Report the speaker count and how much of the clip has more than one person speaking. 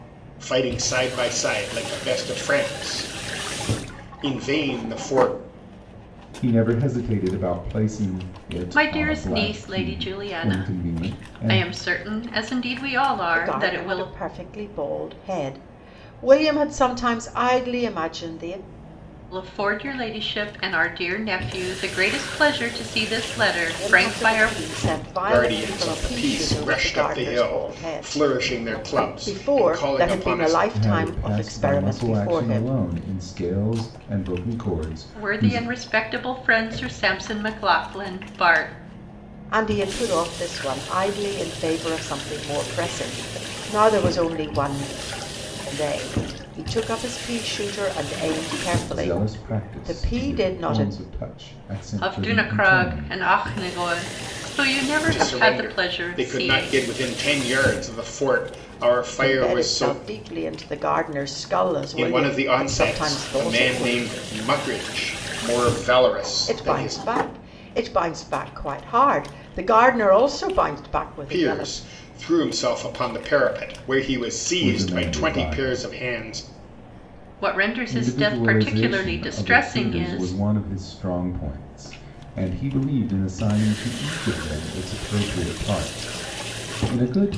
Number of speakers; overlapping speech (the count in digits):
4, about 29%